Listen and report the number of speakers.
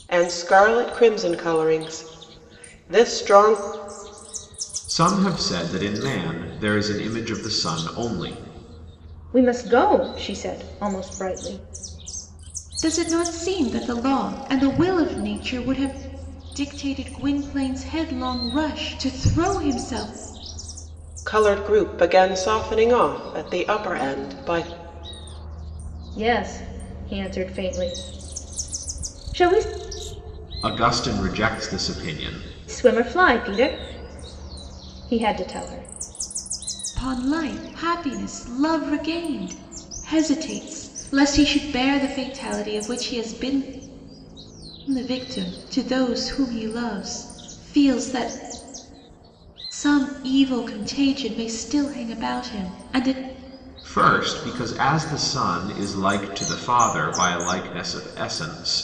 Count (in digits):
4